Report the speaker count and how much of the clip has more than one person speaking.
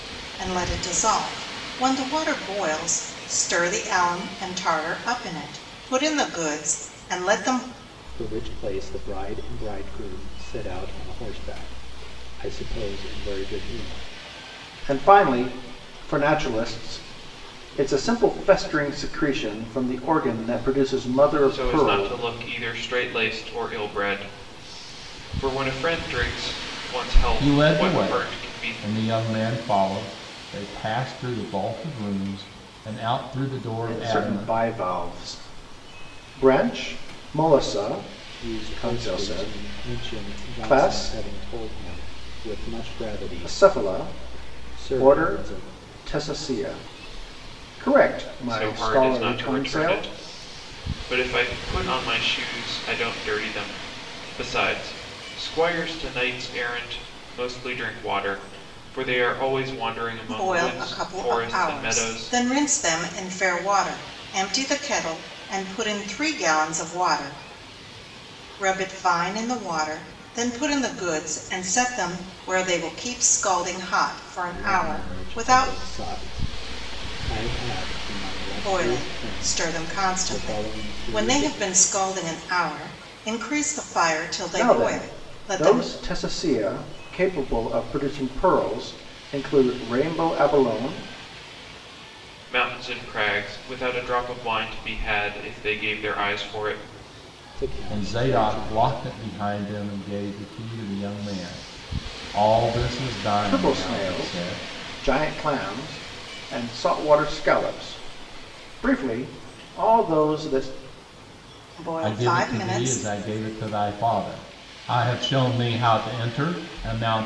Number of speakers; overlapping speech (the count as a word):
five, about 17%